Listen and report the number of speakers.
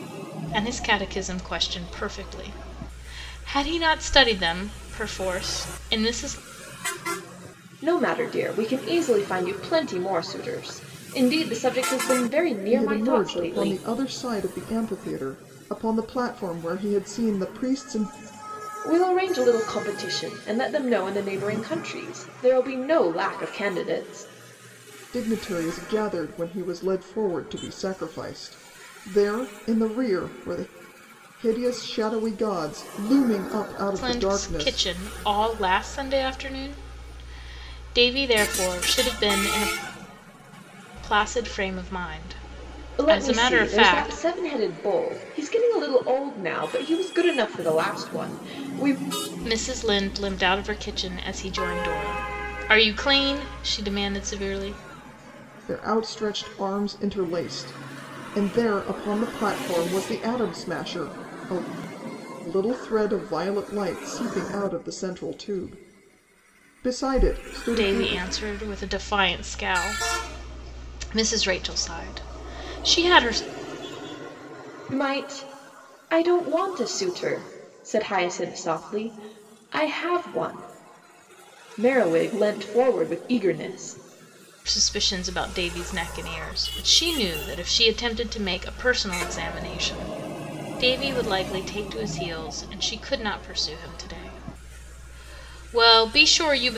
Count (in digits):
3